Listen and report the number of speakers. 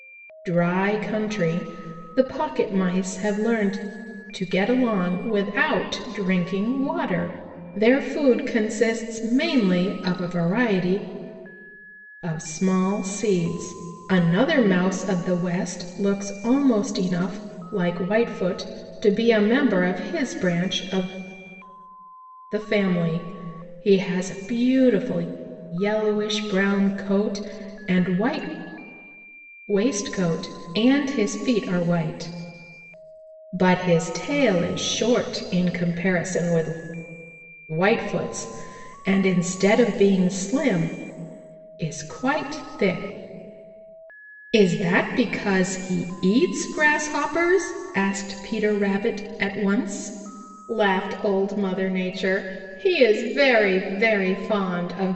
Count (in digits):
1